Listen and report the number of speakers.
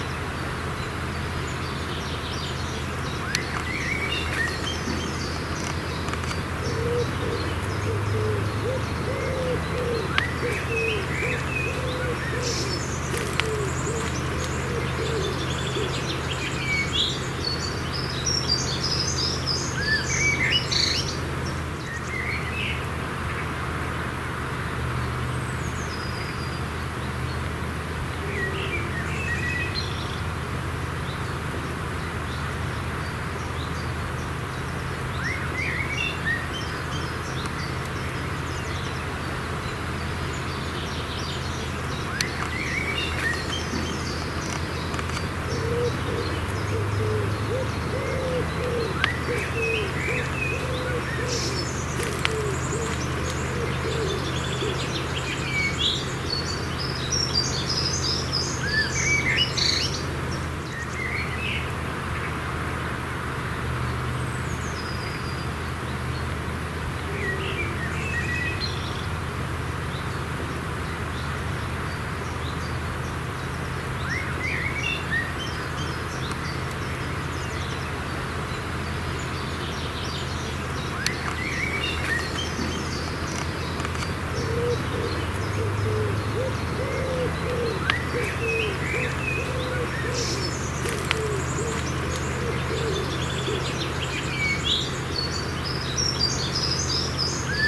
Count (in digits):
0